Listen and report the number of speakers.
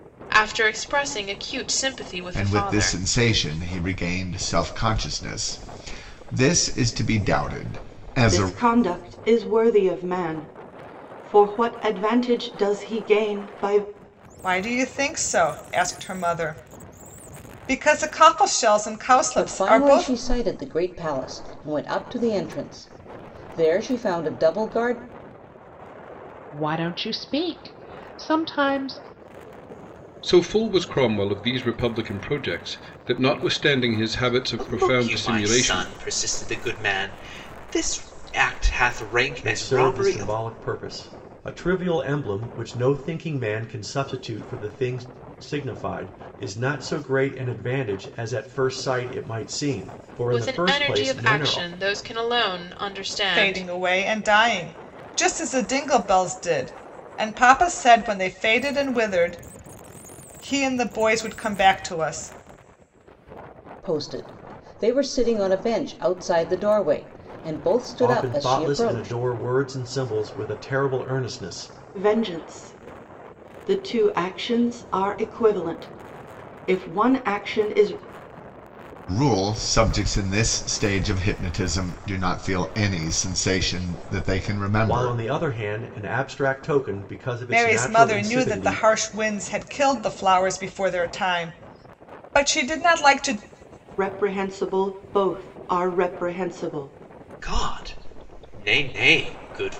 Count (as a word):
nine